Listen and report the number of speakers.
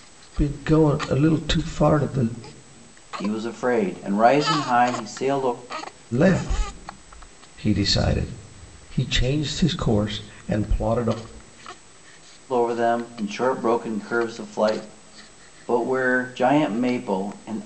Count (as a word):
two